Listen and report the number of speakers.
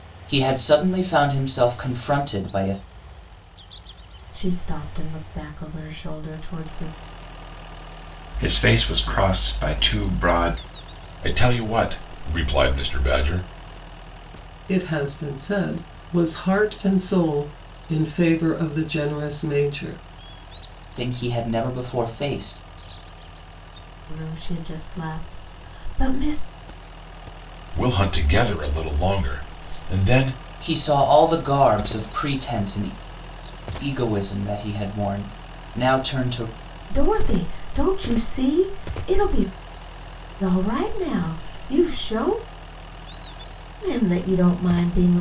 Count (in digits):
5